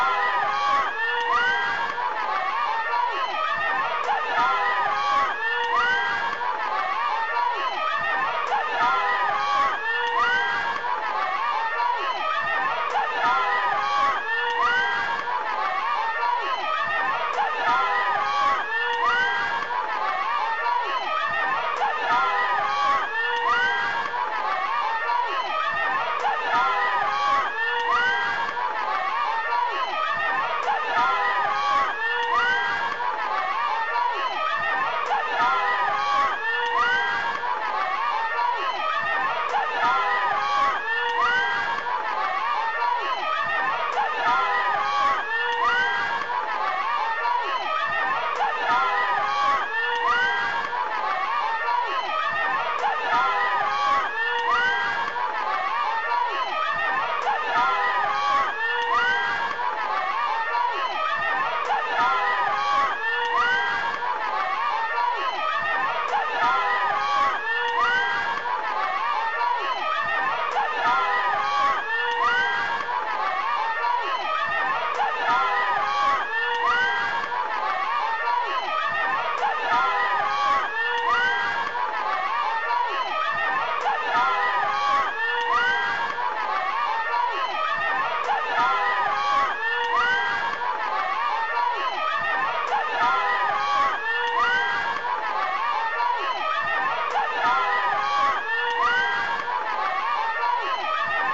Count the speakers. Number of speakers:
zero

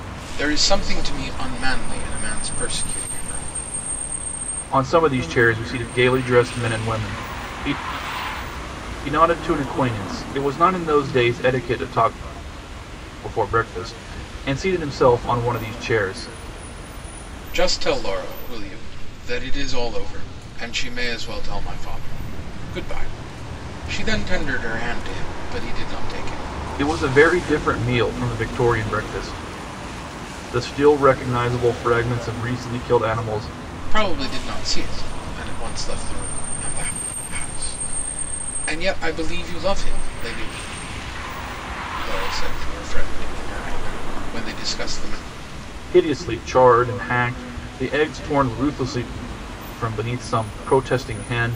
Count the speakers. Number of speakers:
two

